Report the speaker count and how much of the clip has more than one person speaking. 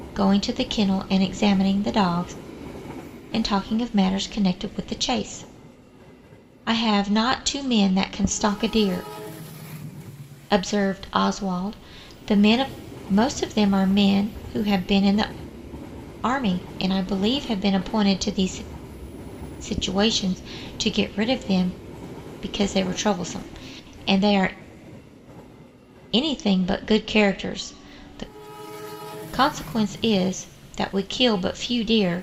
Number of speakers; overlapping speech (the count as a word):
one, no overlap